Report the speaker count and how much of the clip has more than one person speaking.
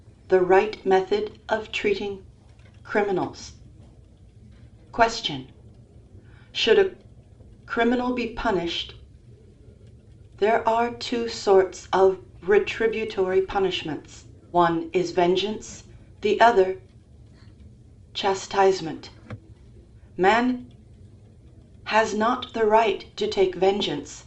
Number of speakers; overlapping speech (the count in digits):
1, no overlap